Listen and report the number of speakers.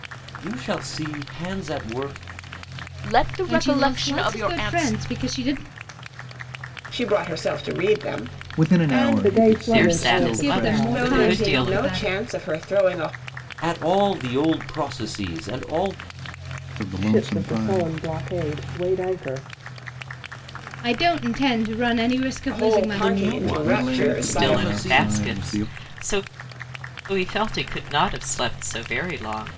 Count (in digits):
7